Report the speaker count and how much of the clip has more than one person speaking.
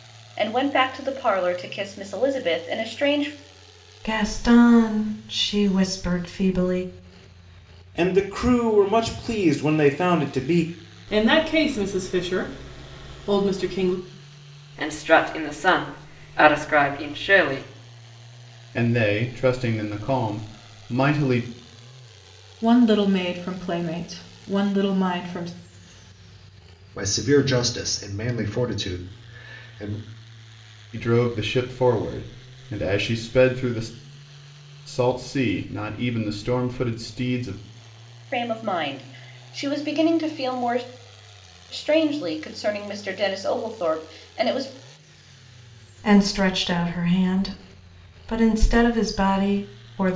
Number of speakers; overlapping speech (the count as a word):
eight, no overlap